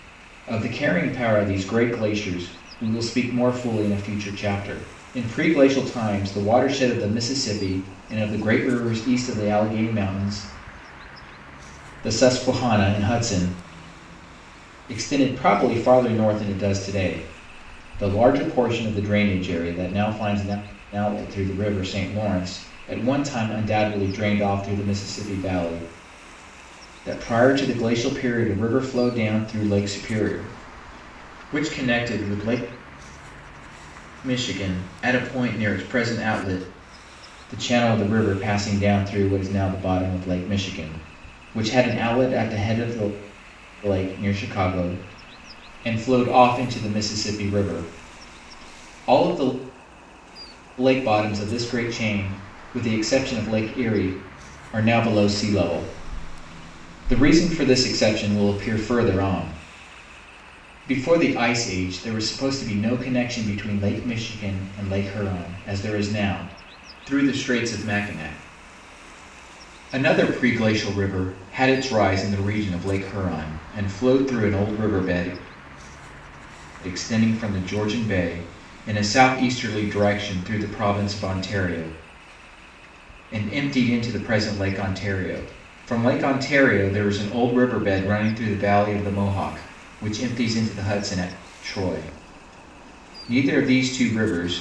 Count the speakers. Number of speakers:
1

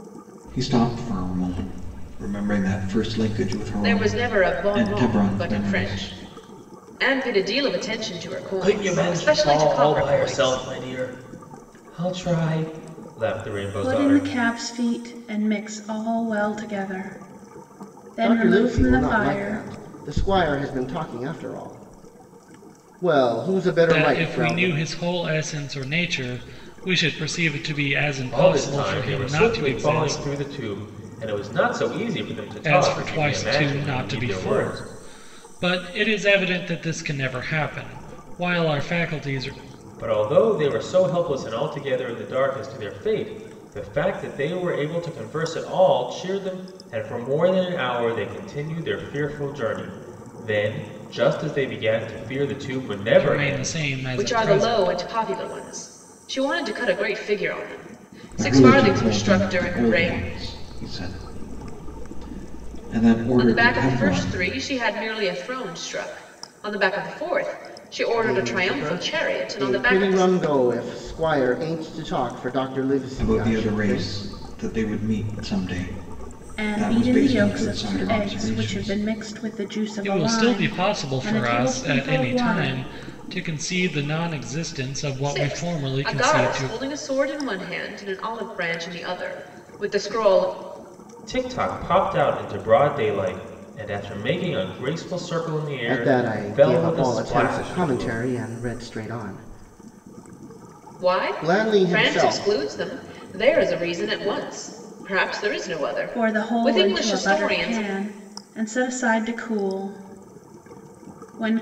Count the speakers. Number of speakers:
6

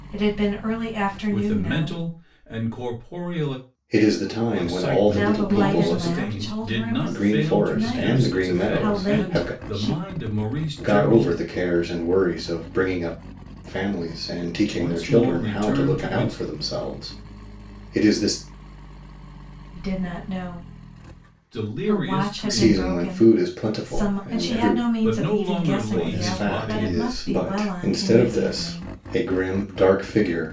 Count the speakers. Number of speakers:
3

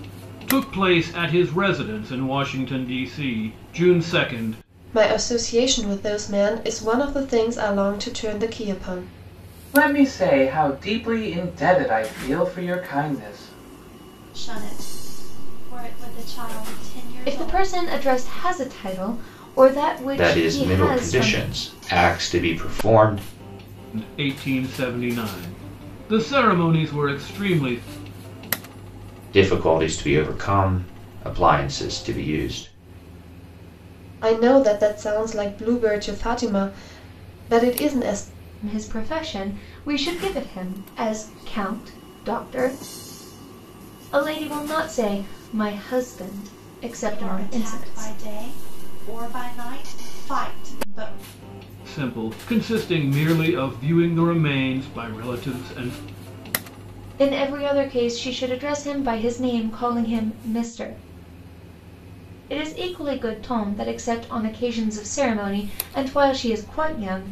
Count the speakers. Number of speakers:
6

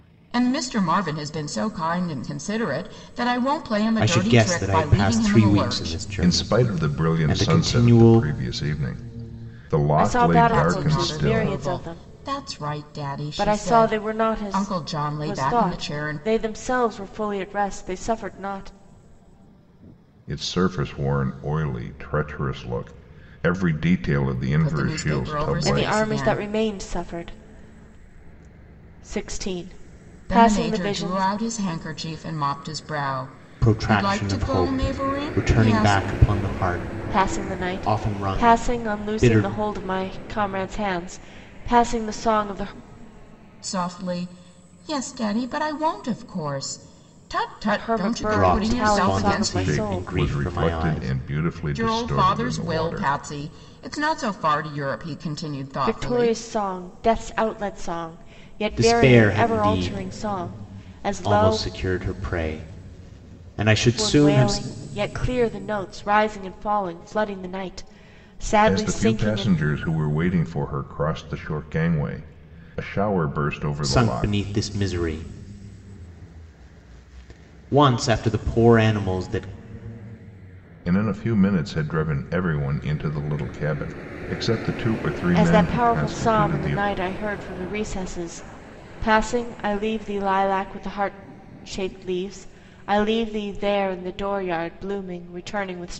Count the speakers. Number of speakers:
4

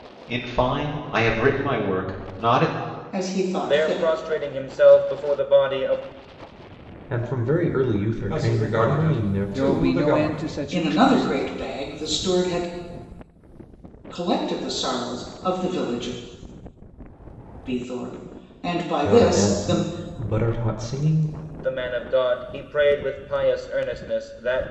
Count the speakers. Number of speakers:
6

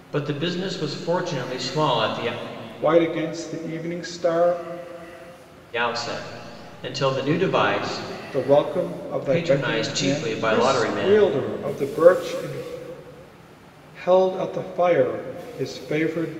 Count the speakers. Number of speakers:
2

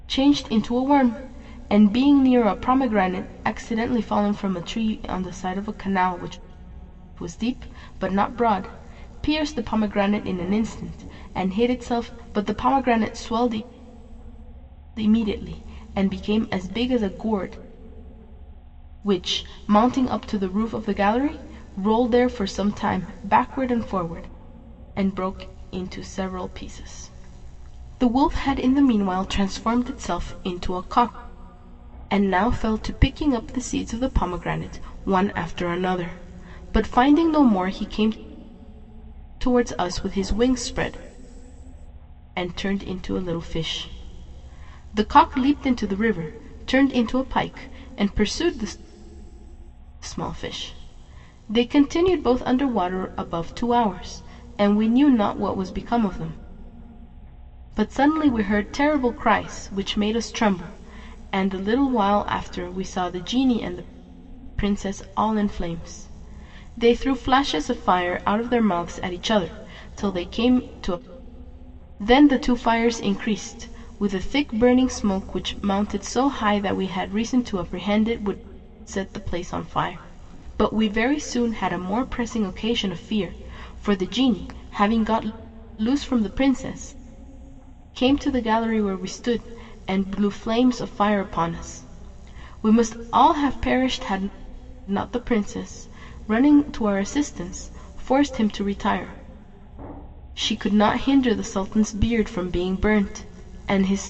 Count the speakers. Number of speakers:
1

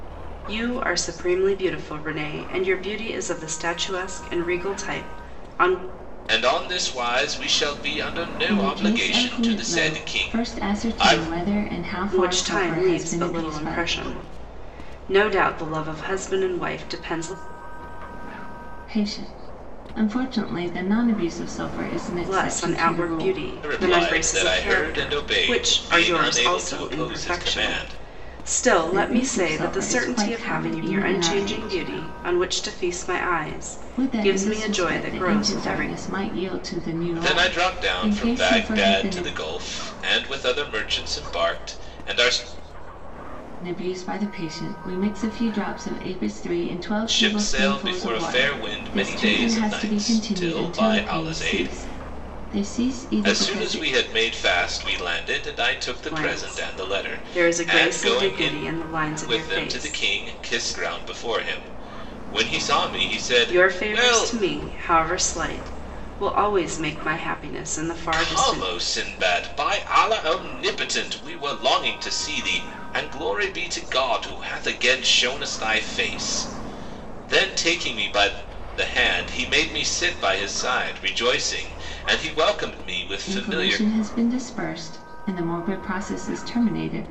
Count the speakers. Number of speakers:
3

